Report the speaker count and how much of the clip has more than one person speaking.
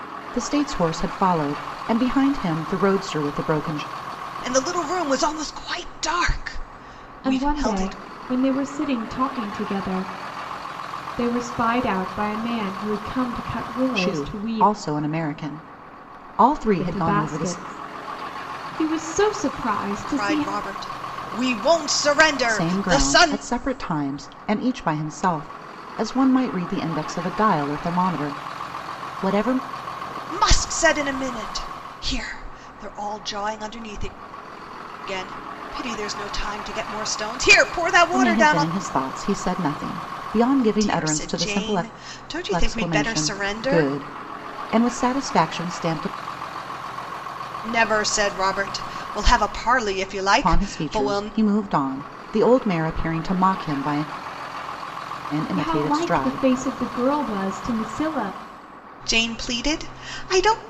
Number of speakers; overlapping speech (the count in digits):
3, about 15%